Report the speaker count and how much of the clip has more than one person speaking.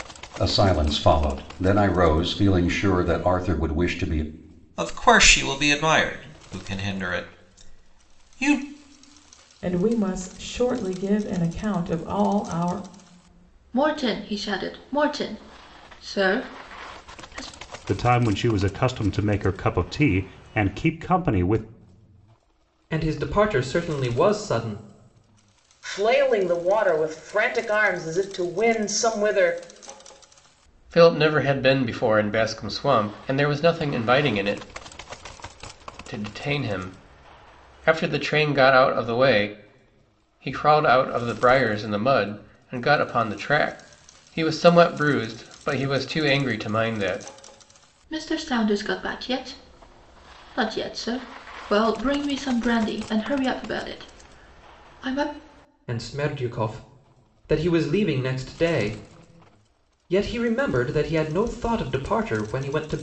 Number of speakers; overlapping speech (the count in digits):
8, no overlap